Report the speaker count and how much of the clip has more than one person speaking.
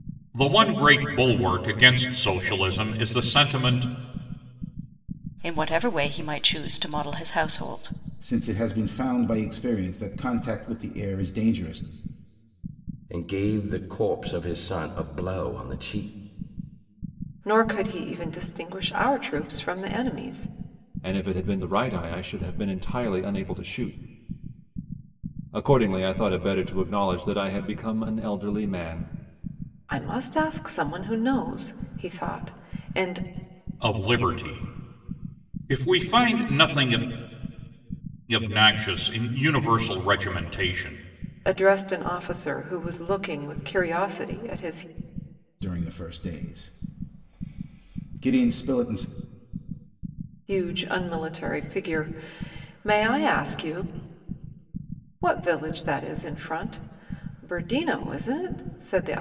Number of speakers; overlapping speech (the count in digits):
6, no overlap